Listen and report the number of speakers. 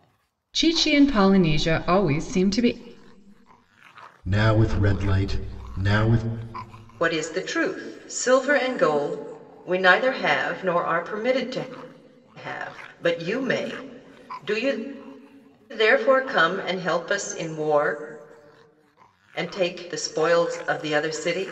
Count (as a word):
three